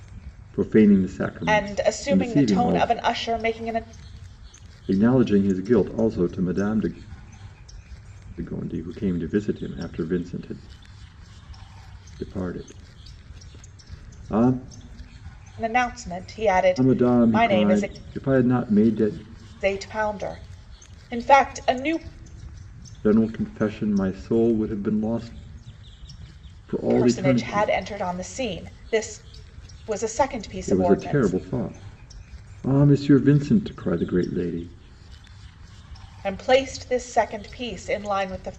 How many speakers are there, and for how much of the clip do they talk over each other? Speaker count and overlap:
2, about 11%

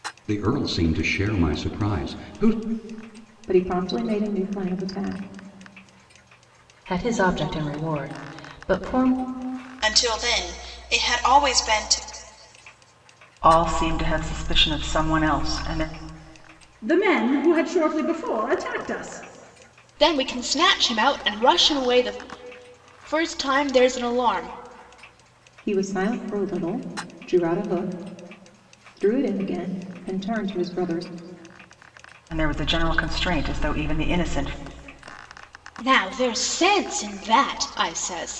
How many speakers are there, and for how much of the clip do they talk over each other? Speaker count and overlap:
7, no overlap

